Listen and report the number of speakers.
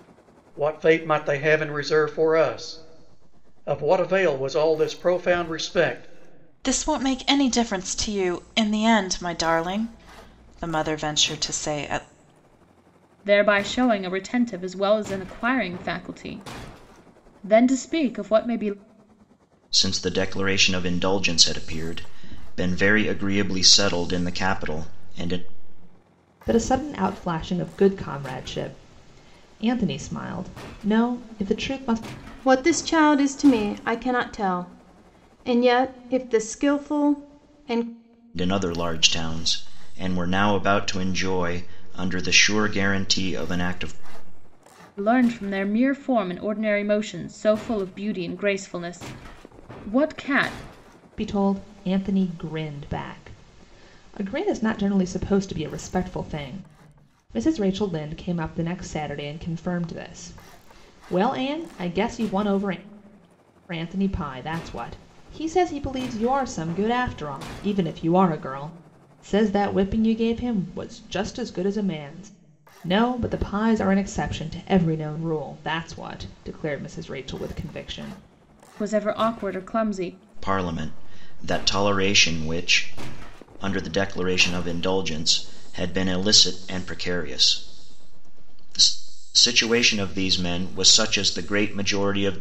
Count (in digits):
6